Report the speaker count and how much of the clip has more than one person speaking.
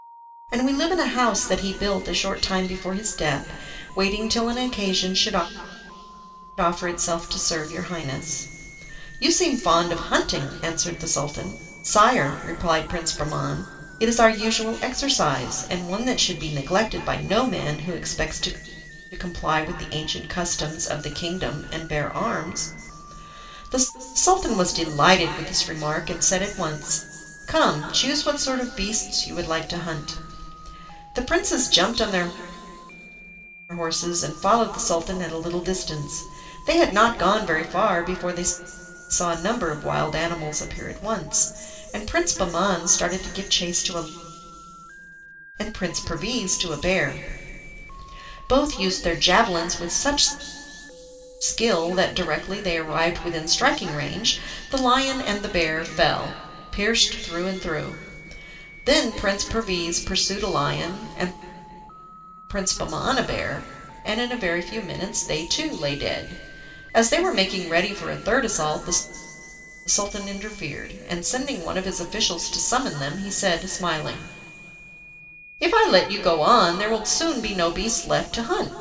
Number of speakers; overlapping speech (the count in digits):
1, no overlap